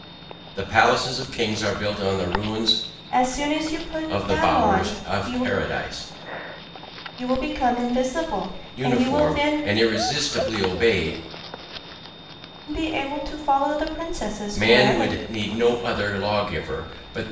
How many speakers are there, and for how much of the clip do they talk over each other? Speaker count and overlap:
2, about 17%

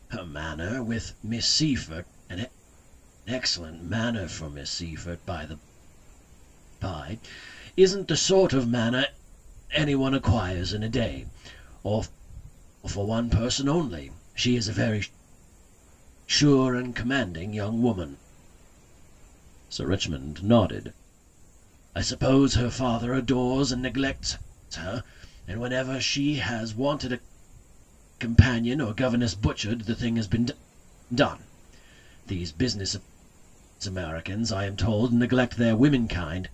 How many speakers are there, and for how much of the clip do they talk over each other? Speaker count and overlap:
1, no overlap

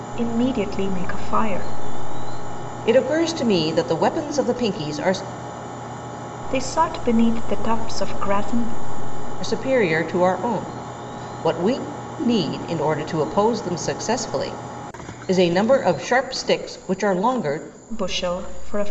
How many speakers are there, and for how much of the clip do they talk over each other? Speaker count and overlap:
2, no overlap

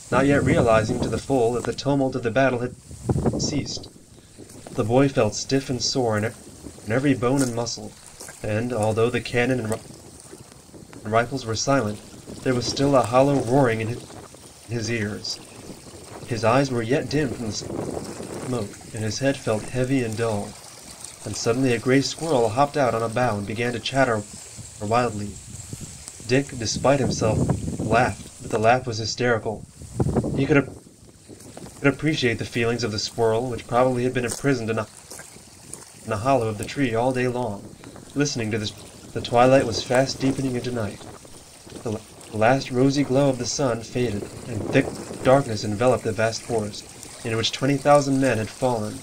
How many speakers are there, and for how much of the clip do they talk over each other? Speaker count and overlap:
1, no overlap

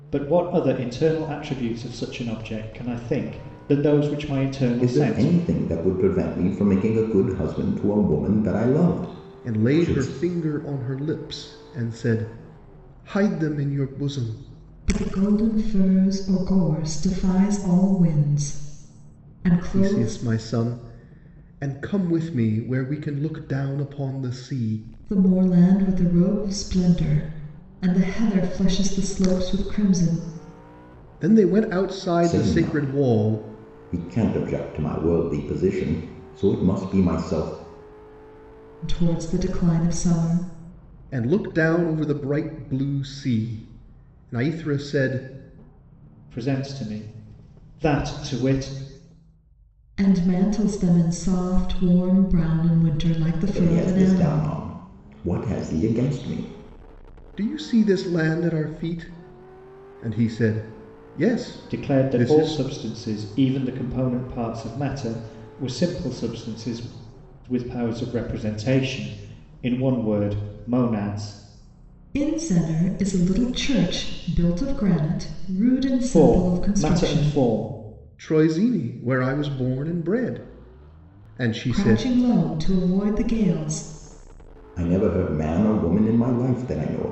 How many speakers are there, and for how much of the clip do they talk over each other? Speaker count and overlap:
4, about 8%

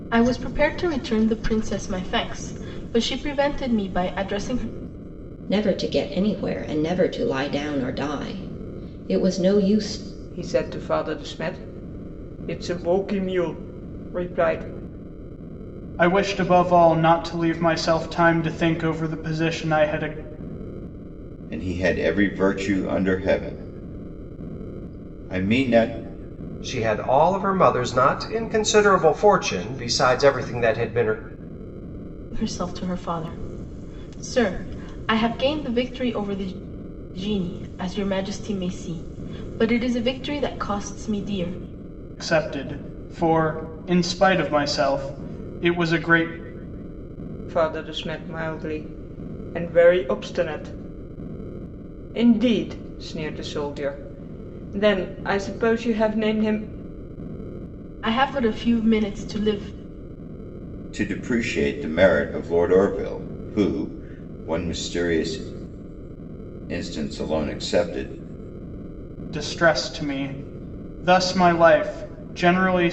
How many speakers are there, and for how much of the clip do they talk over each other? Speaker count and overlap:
6, no overlap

